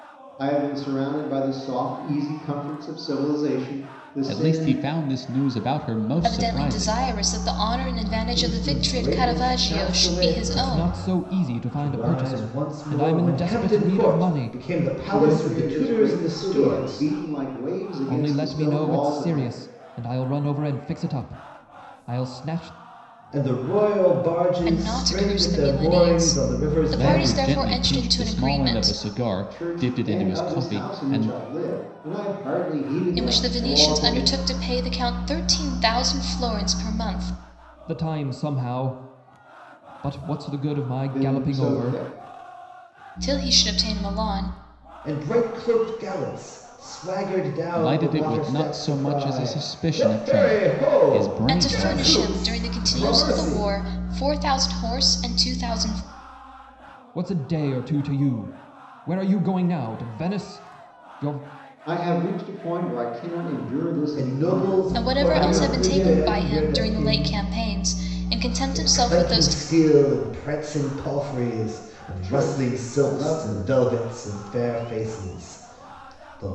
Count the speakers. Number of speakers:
5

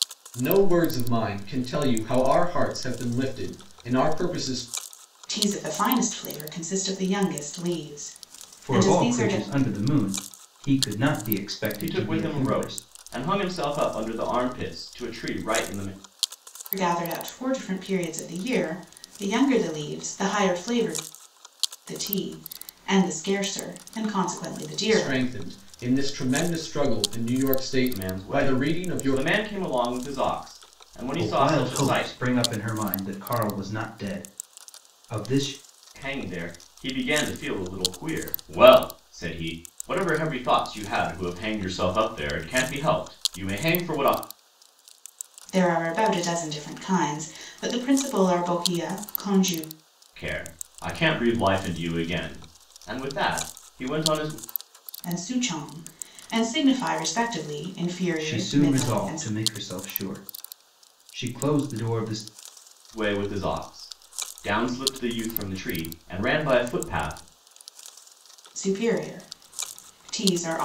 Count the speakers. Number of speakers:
4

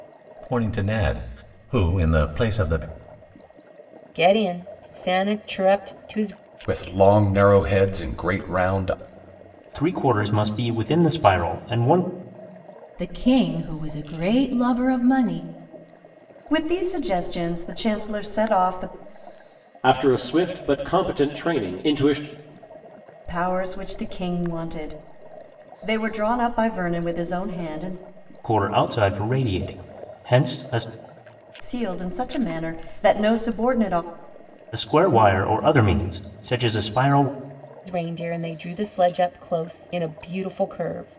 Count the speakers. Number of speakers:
7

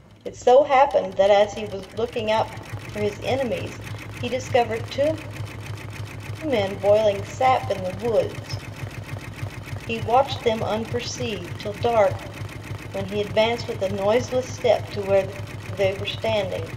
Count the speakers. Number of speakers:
1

